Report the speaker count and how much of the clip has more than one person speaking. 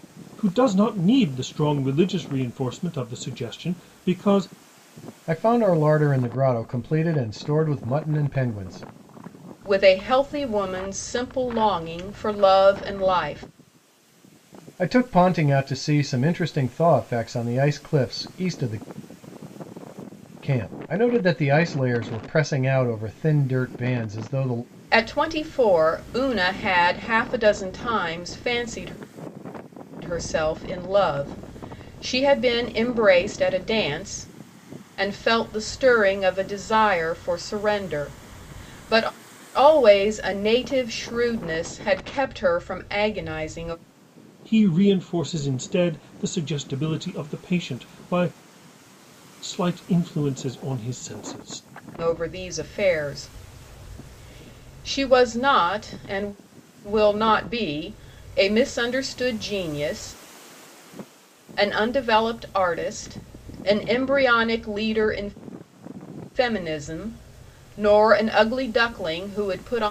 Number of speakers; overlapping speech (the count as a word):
three, no overlap